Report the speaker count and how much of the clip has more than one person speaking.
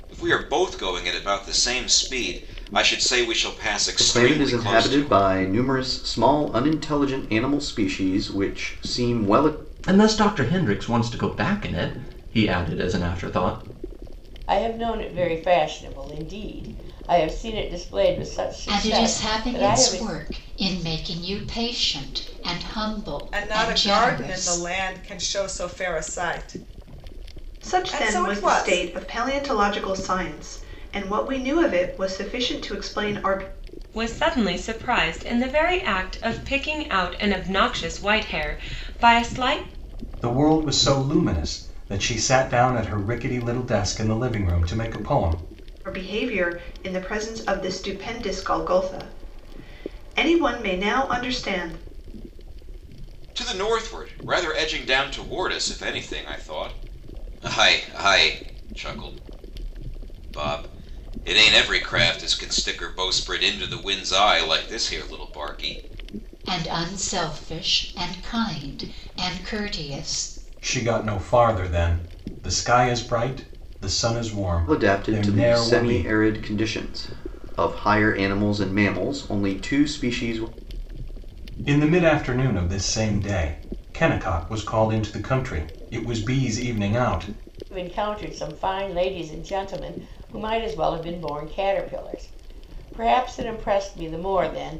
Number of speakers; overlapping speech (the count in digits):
9, about 7%